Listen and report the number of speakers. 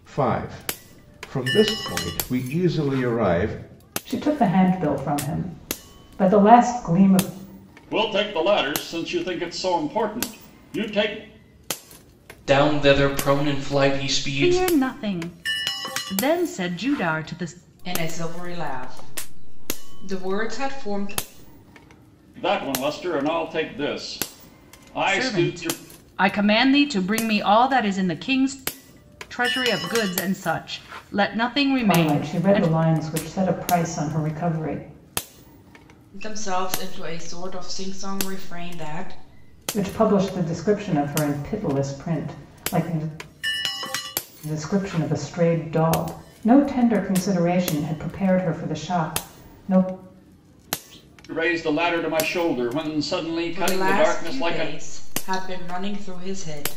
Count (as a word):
six